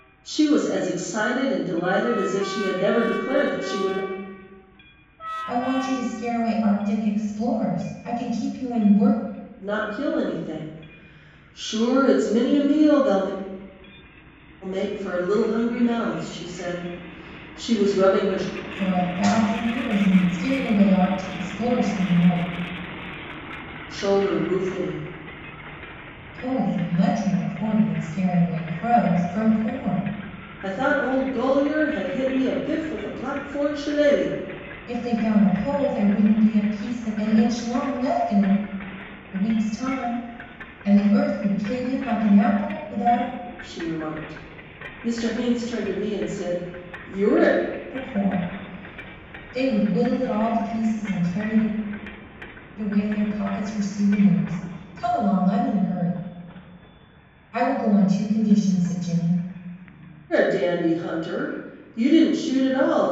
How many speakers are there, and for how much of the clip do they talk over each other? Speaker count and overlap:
2, no overlap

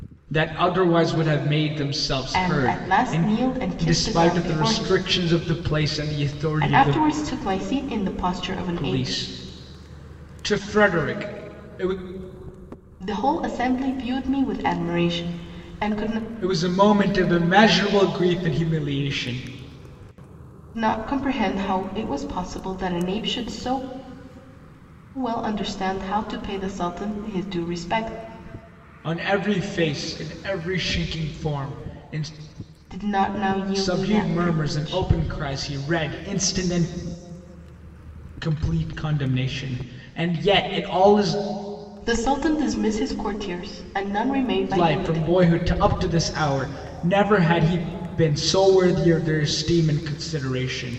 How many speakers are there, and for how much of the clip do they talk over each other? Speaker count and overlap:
2, about 10%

